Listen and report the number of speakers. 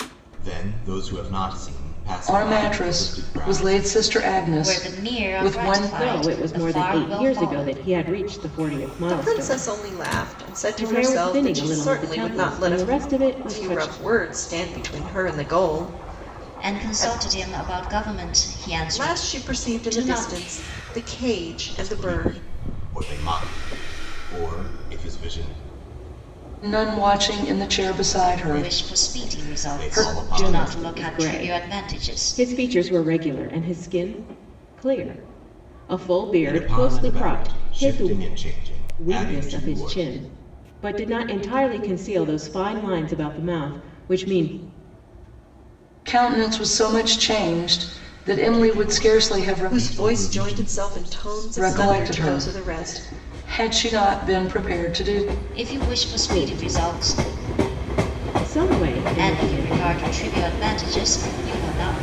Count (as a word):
five